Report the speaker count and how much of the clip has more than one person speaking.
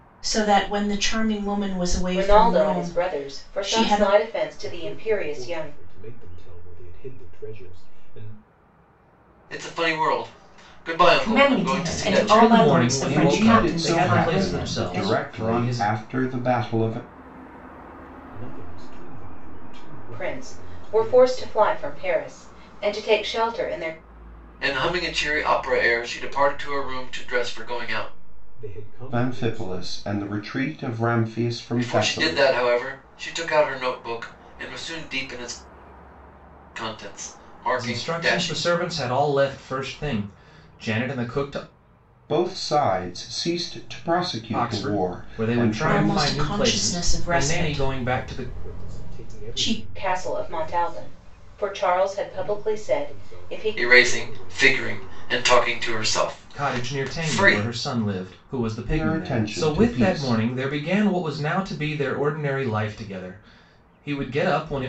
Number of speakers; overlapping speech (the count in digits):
7, about 43%